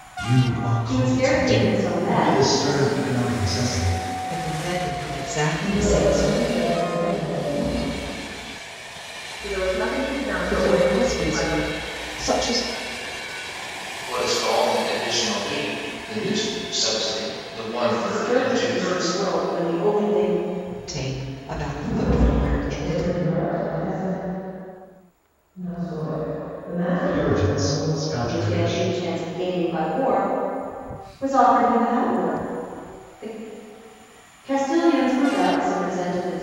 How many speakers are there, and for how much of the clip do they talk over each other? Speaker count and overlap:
8, about 22%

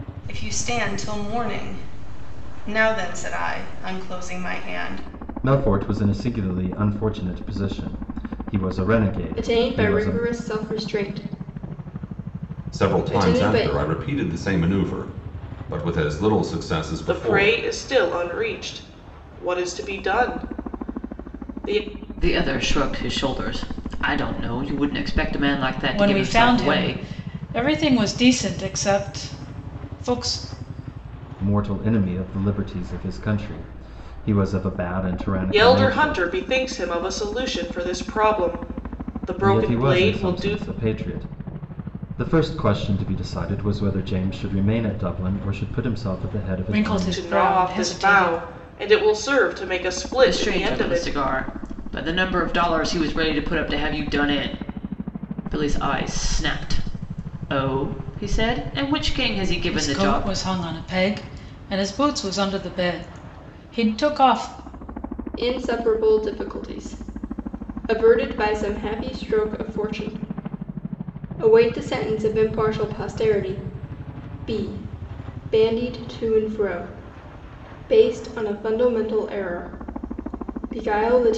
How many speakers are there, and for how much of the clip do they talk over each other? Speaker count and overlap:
7, about 11%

